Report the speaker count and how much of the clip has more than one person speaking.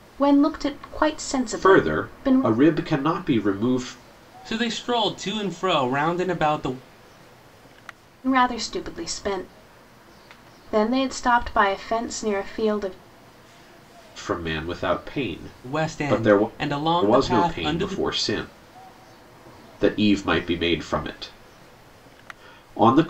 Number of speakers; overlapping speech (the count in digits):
3, about 12%